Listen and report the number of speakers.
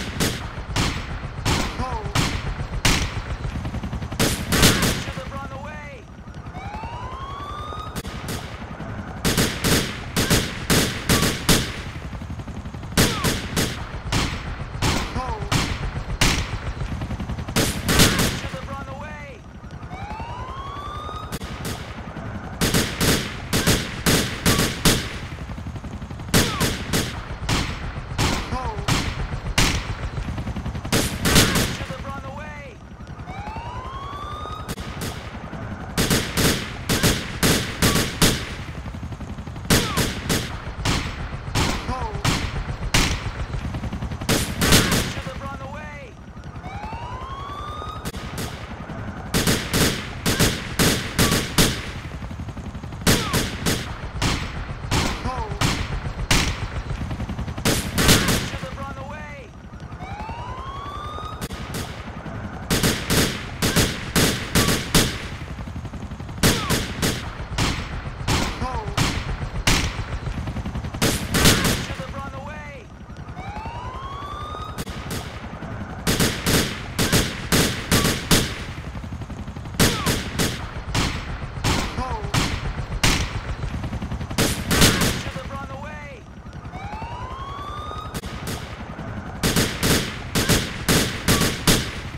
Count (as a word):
zero